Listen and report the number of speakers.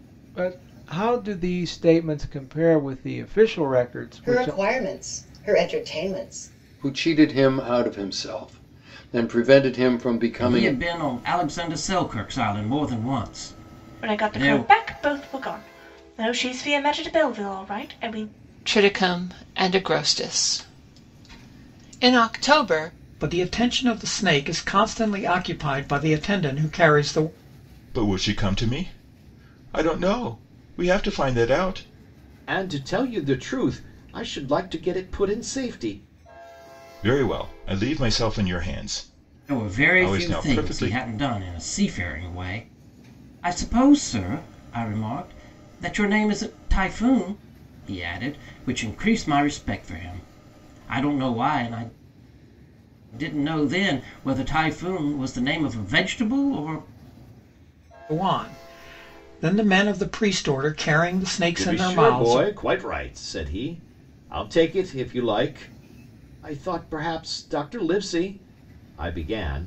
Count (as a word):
nine